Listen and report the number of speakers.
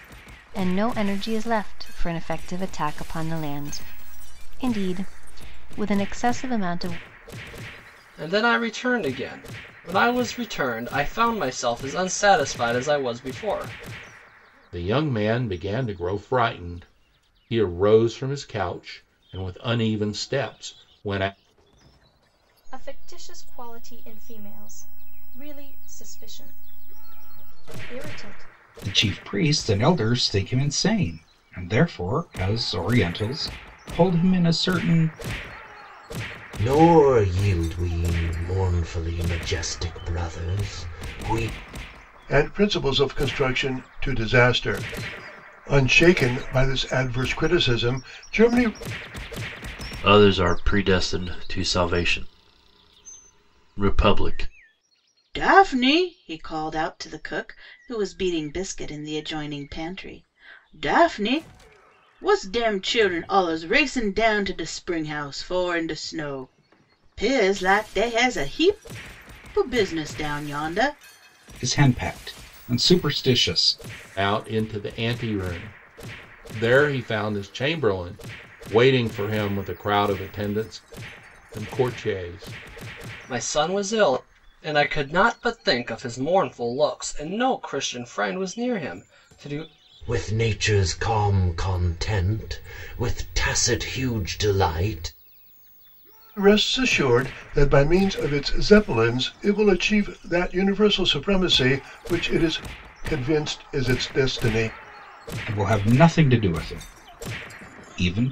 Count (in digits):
9